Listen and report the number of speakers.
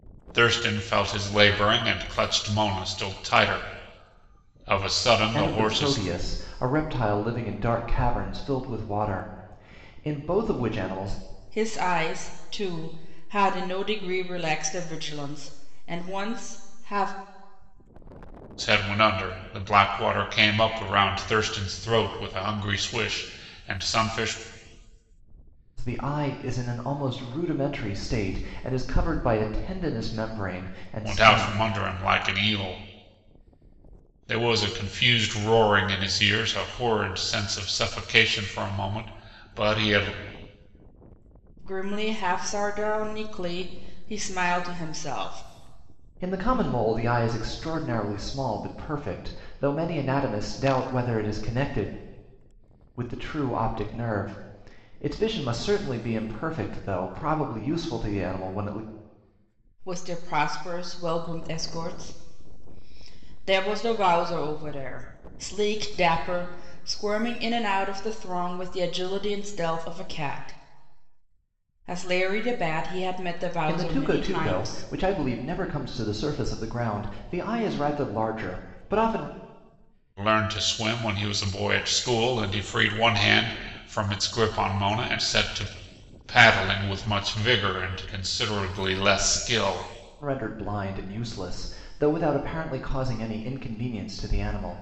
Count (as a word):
three